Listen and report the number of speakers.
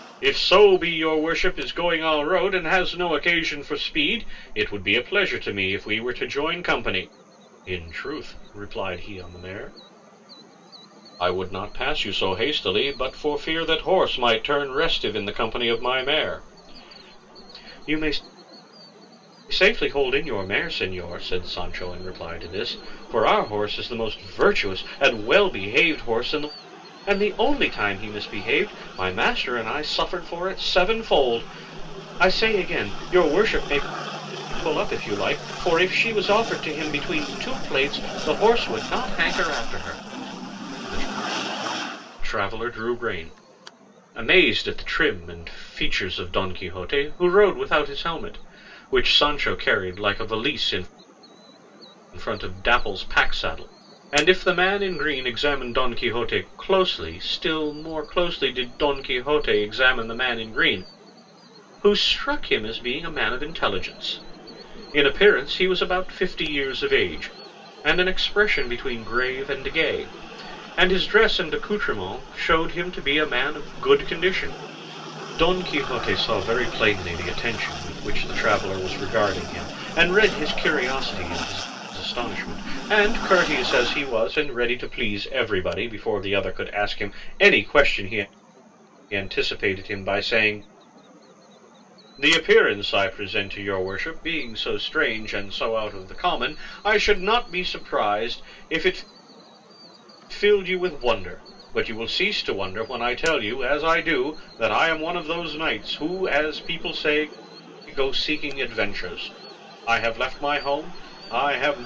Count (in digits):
1